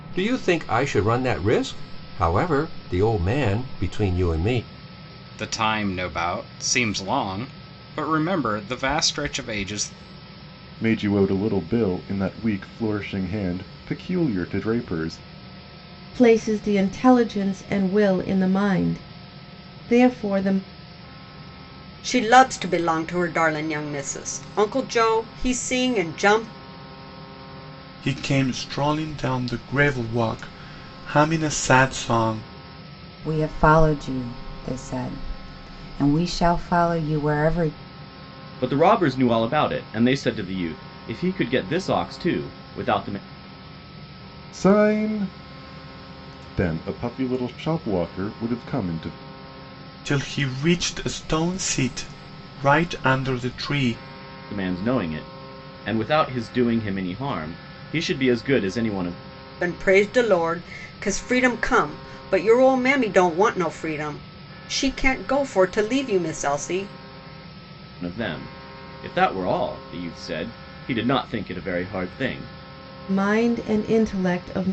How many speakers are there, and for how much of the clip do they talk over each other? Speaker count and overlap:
eight, no overlap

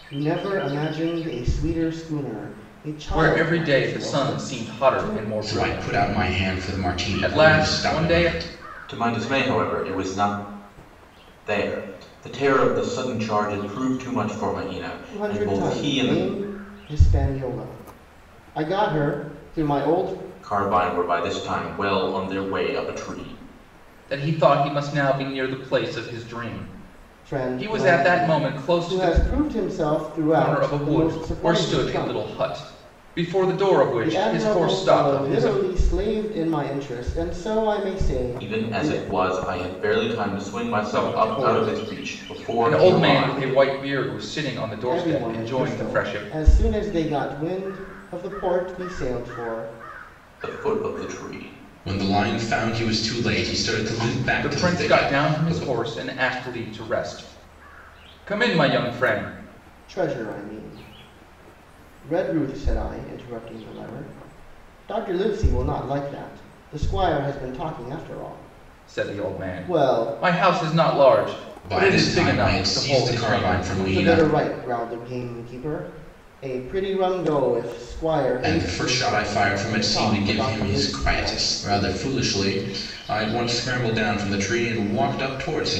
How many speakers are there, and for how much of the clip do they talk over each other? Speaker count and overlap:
three, about 29%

